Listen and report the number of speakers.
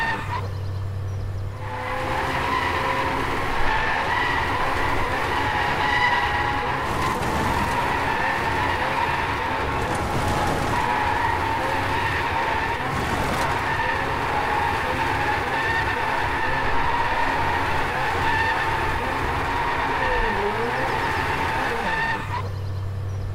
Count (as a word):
zero